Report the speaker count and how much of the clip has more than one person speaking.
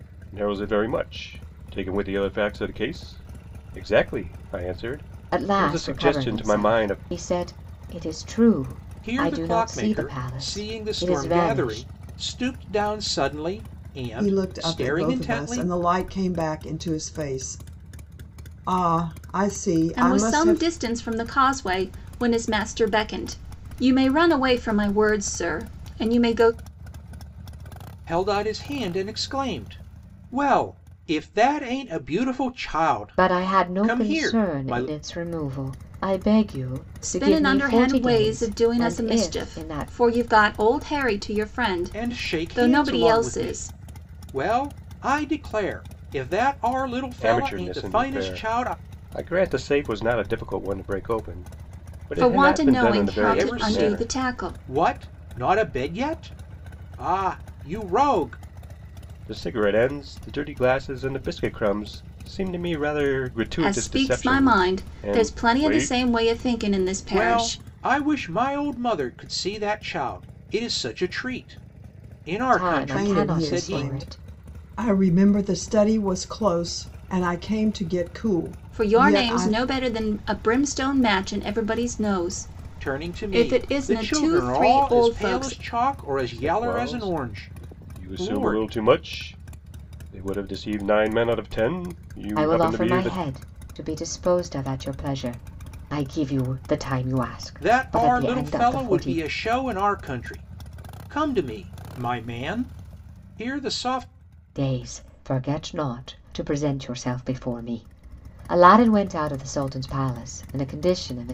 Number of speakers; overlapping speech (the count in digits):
5, about 28%